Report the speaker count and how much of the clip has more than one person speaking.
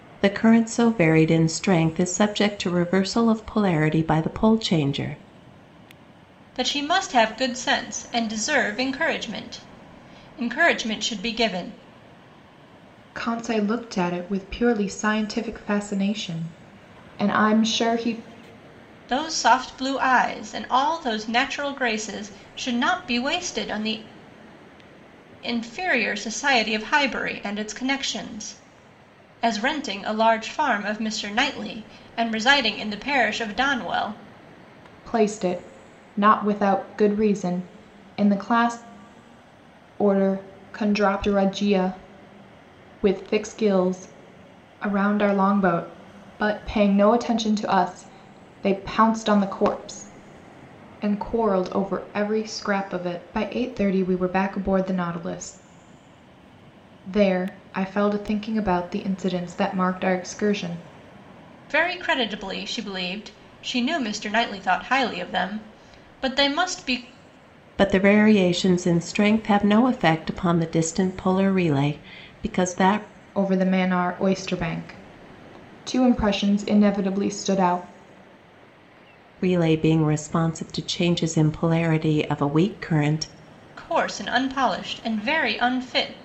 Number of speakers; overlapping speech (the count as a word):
three, no overlap